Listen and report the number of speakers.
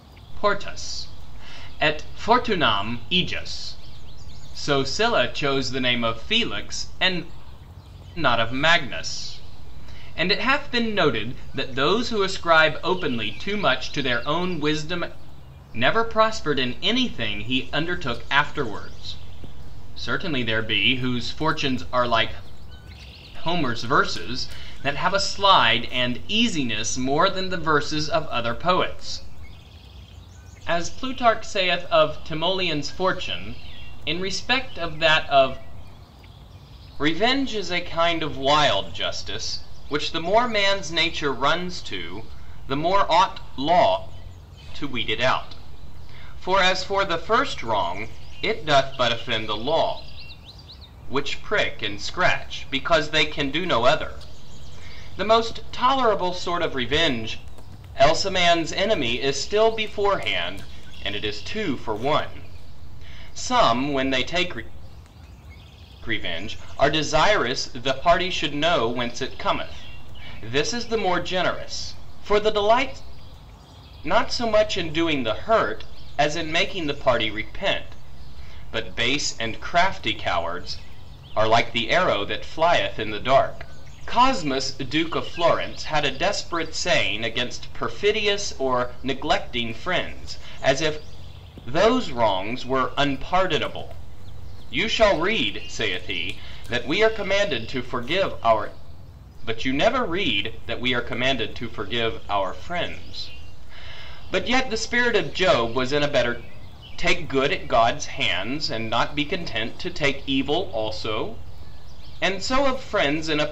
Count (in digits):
1